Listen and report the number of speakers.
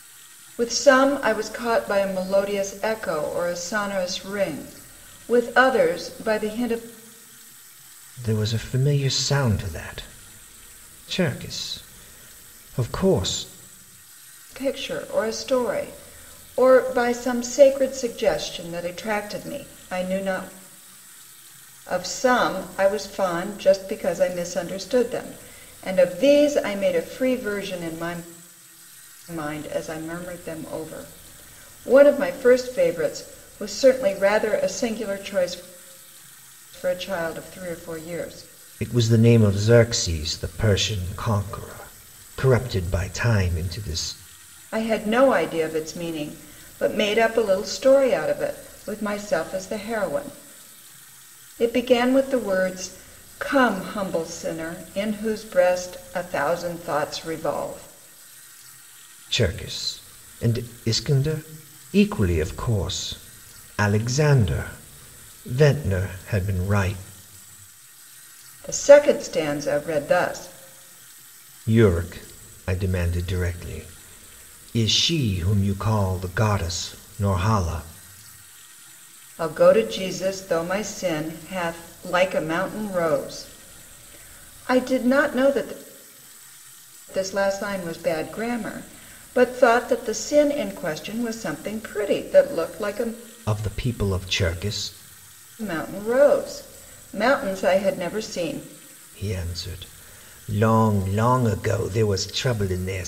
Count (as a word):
two